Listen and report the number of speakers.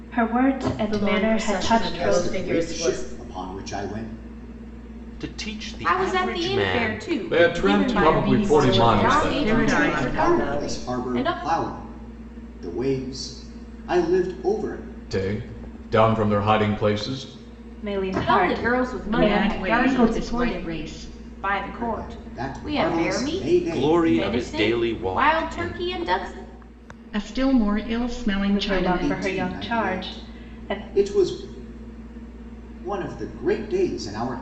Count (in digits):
7